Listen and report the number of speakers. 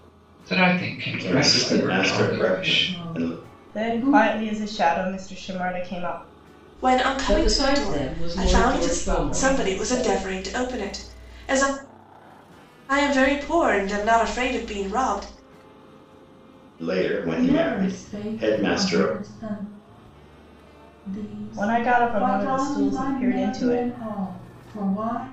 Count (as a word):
six